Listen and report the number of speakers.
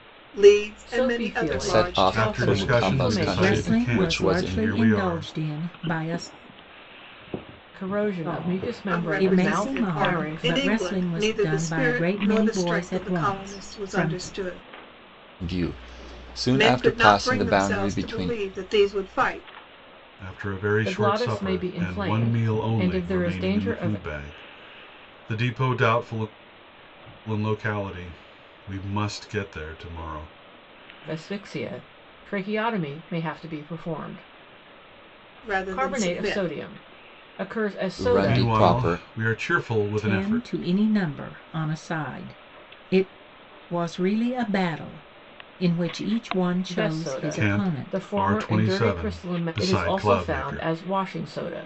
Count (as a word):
five